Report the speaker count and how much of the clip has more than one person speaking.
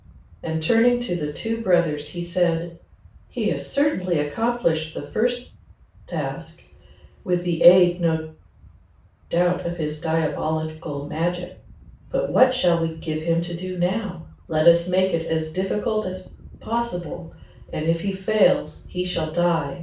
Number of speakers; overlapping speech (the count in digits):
1, no overlap